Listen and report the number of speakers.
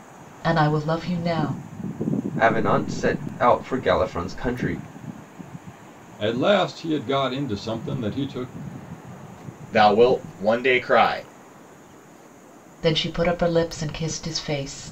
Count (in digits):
4